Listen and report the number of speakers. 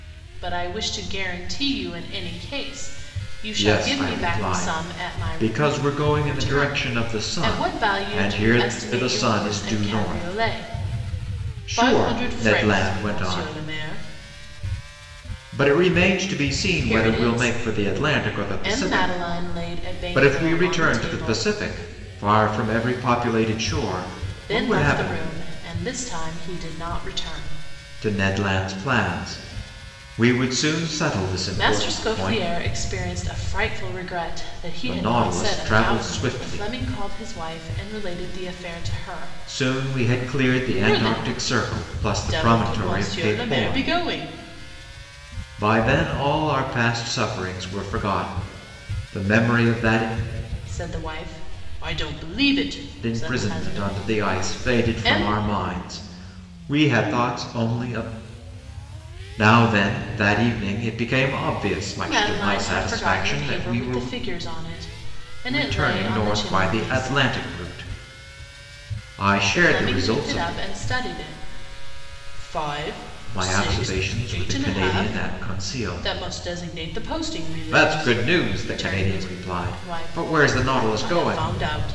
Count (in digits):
2